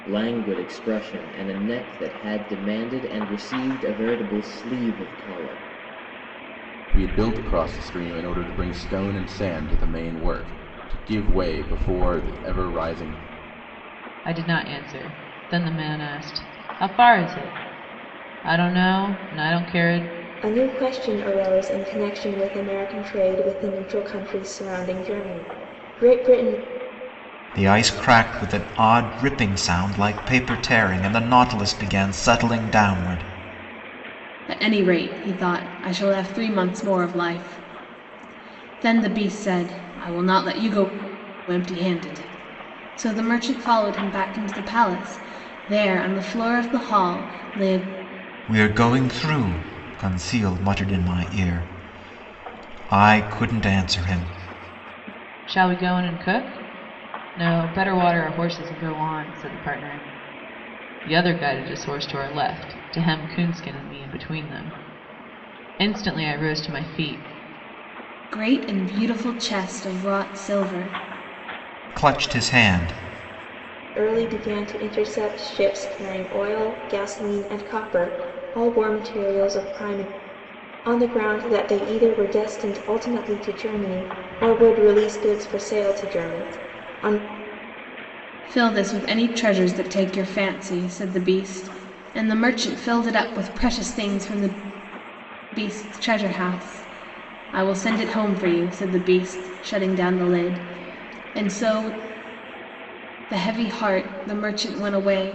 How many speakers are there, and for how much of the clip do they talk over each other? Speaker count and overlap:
six, no overlap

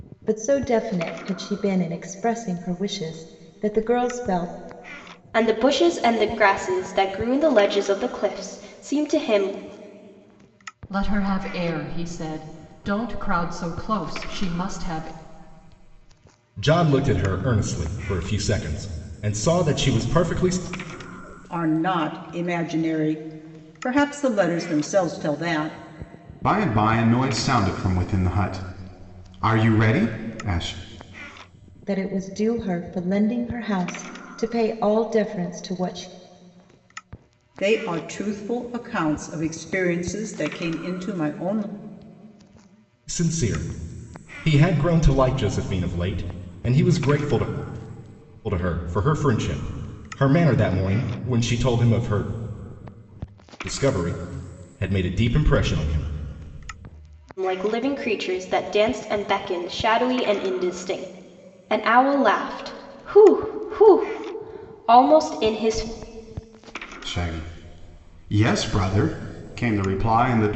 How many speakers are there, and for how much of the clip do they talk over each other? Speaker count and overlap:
six, no overlap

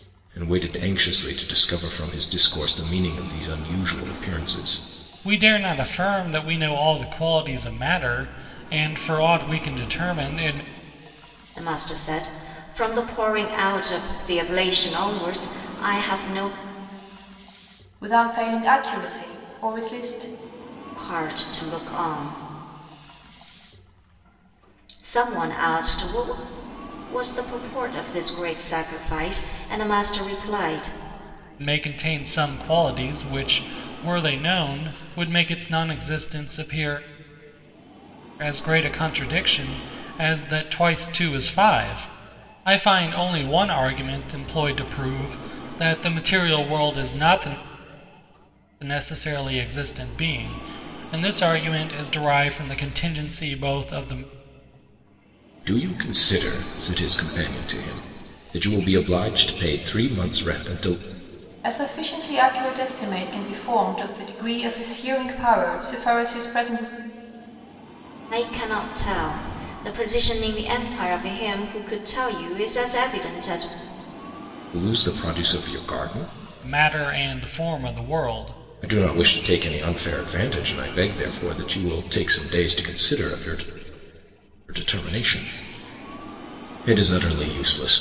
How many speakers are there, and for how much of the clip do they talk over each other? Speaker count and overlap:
four, no overlap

